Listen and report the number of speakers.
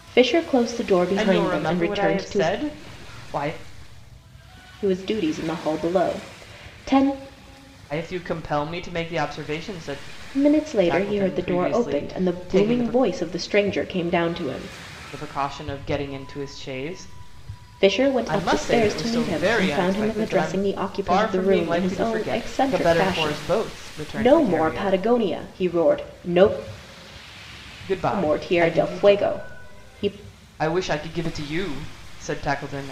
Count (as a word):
two